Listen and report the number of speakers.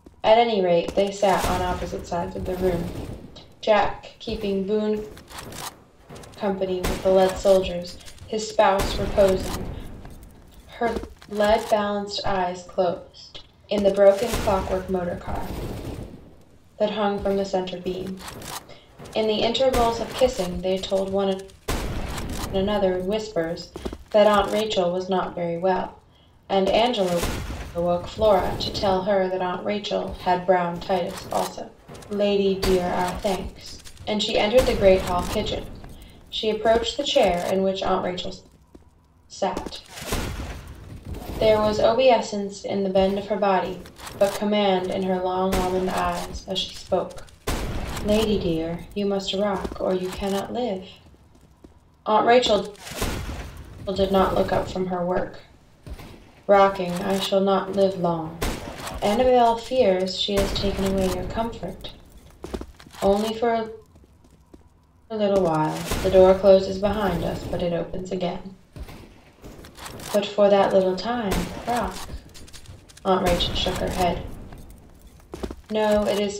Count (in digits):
1